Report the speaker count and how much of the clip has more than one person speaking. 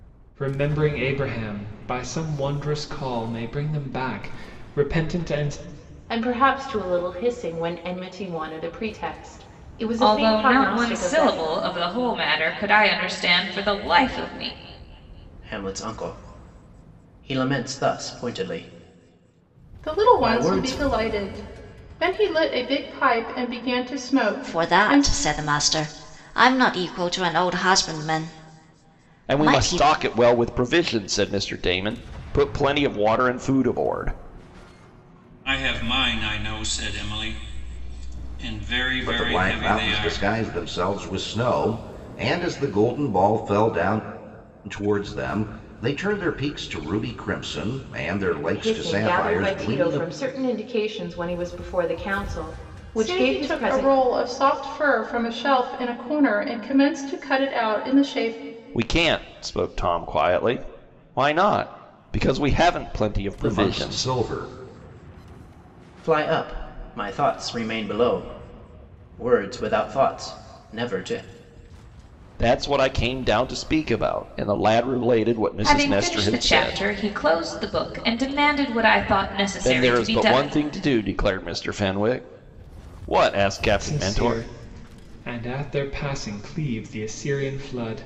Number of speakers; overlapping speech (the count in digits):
9, about 13%